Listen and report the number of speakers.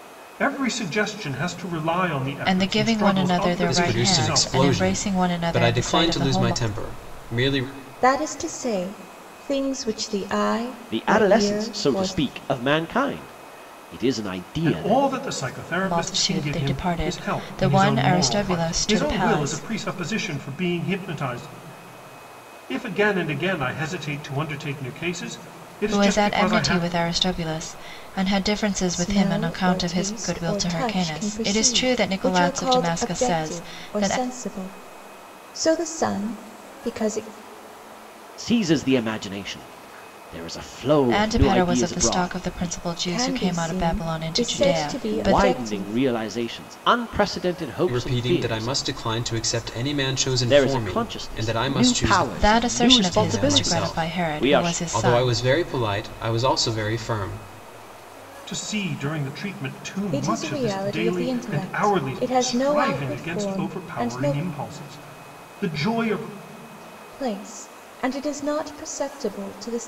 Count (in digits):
5